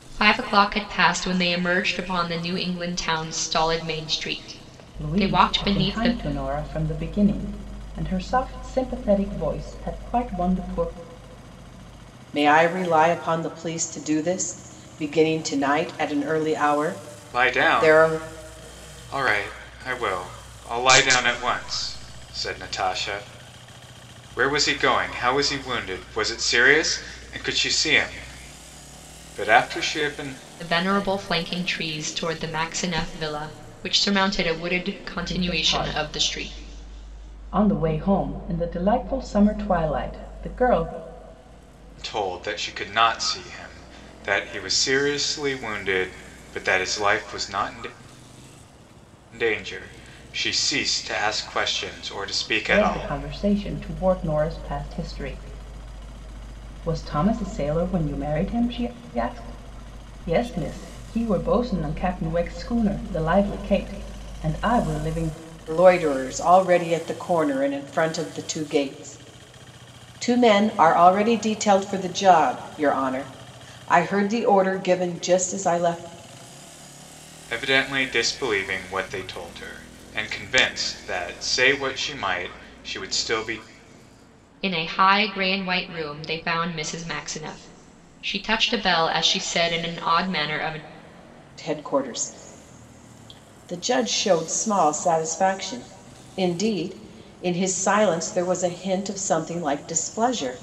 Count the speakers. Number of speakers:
4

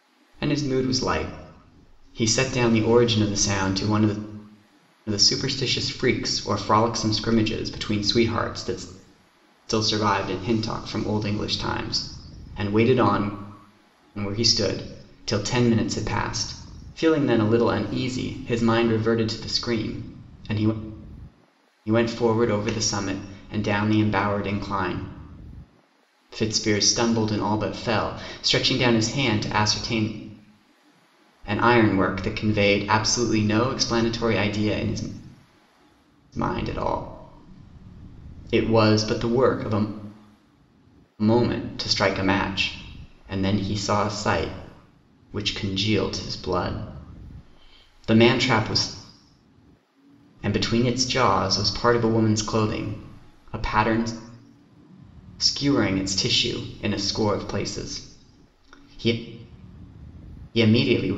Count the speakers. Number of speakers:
1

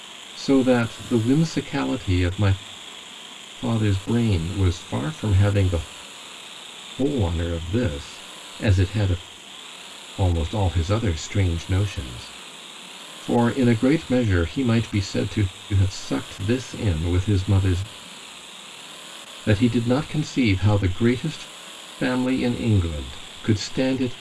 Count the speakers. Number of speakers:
1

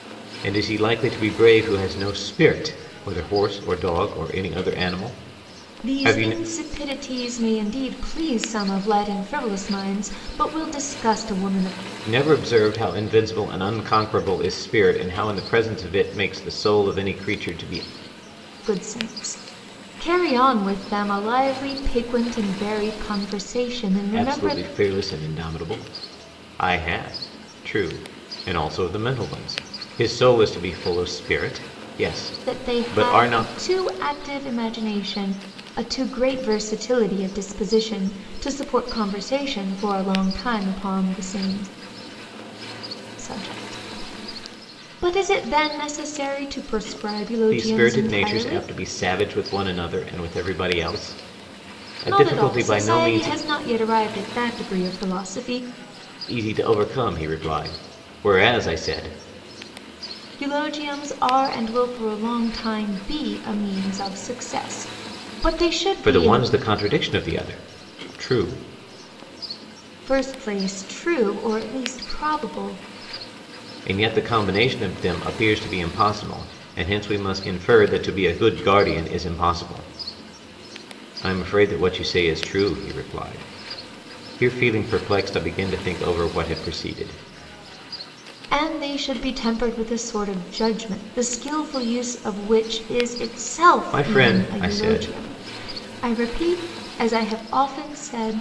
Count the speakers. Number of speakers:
2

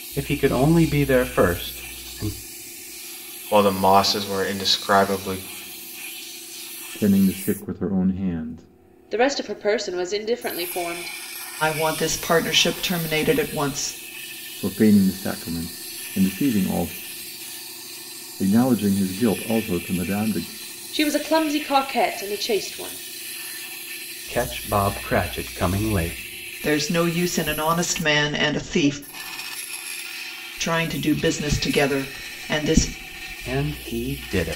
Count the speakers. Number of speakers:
5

